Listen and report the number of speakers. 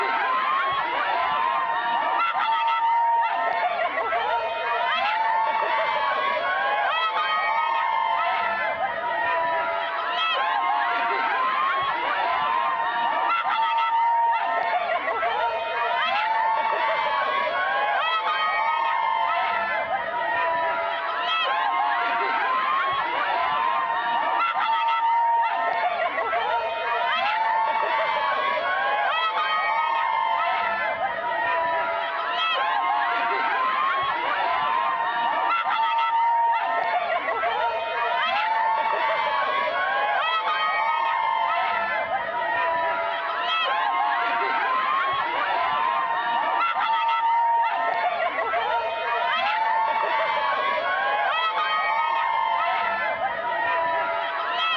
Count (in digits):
0